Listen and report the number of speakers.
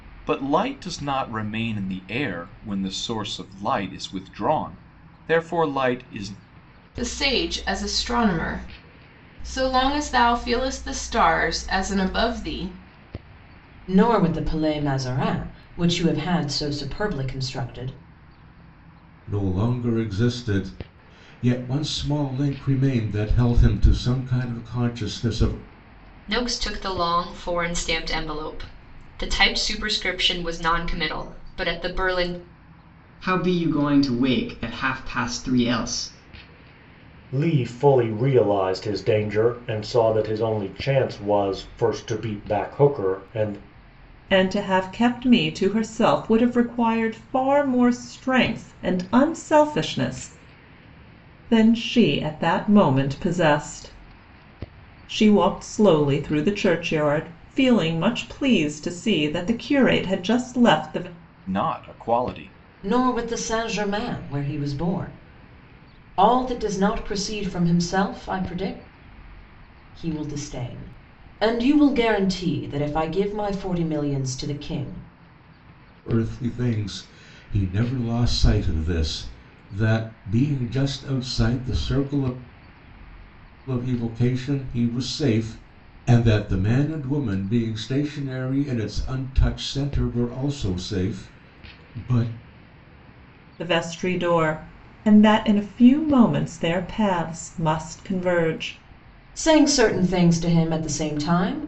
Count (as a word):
eight